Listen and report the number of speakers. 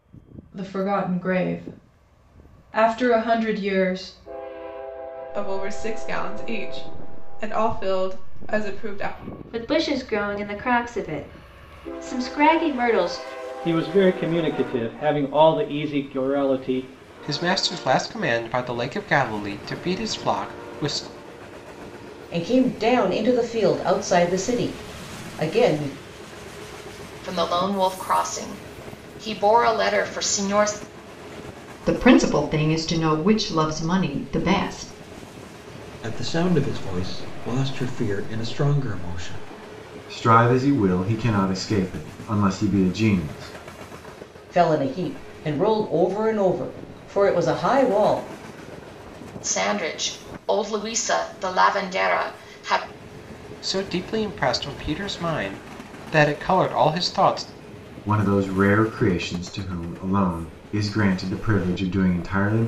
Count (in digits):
10